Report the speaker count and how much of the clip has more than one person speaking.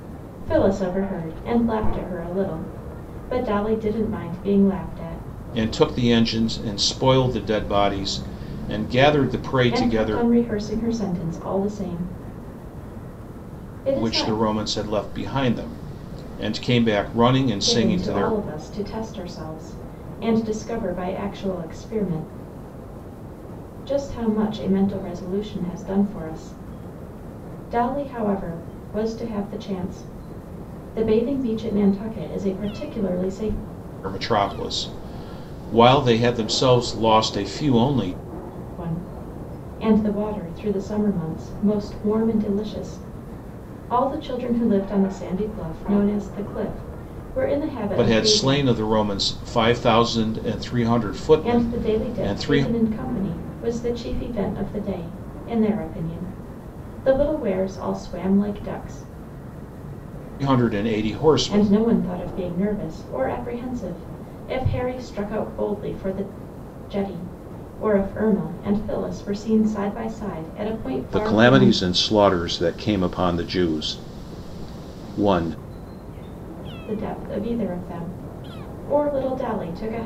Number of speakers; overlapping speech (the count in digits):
2, about 6%